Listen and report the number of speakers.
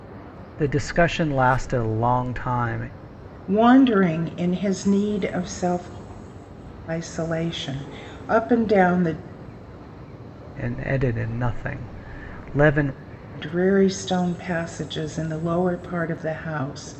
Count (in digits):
2